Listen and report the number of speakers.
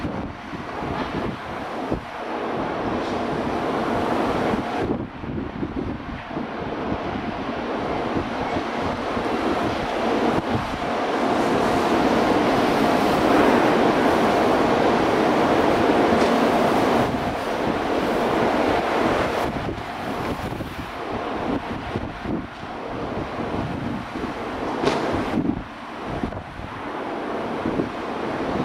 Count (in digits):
0